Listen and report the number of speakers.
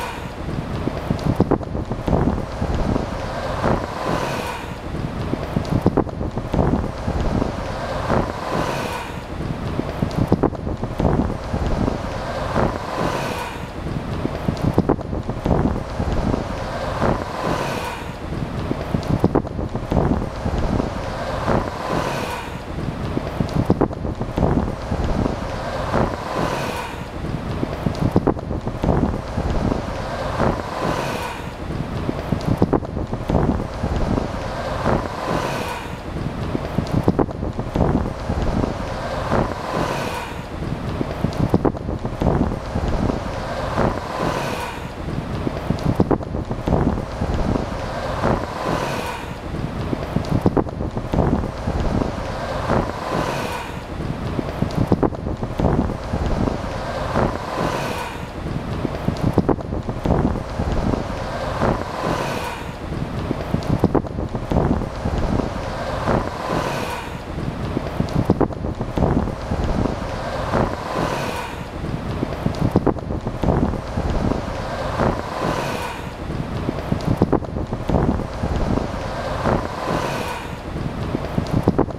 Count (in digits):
0